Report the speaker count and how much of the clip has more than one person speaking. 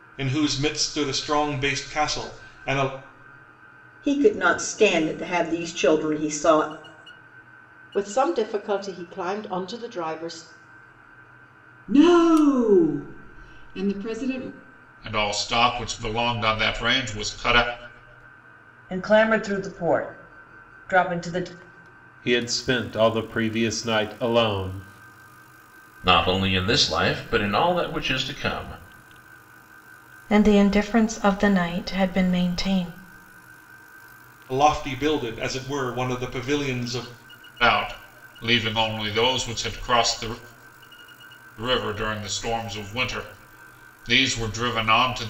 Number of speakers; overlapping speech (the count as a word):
nine, no overlap